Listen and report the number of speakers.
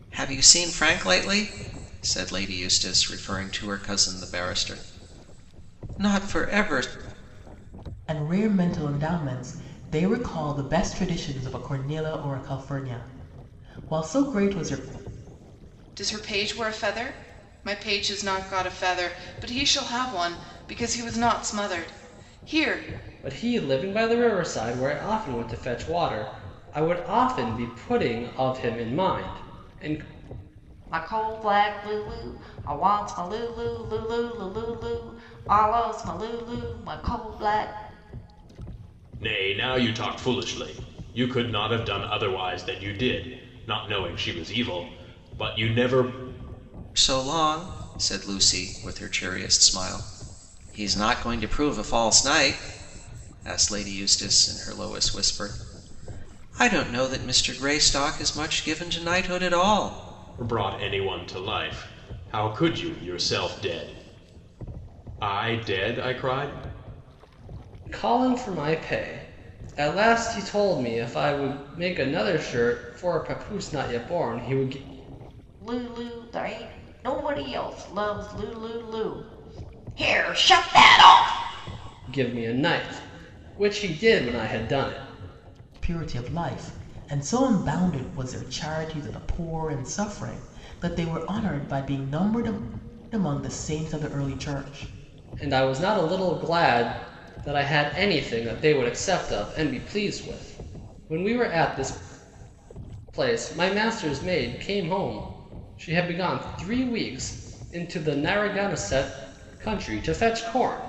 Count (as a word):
six